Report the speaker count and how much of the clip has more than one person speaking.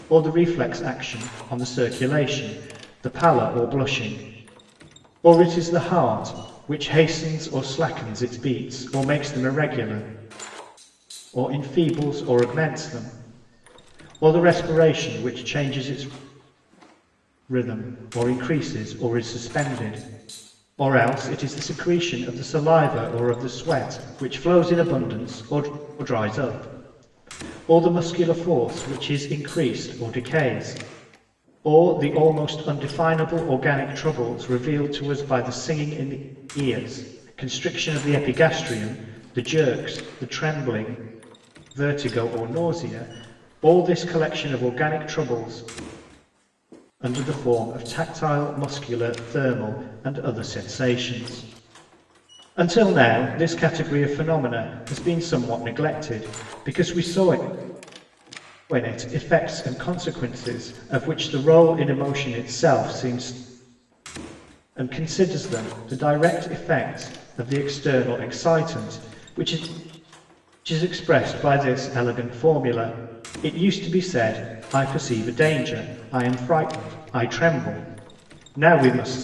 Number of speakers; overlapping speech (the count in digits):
1, no overlap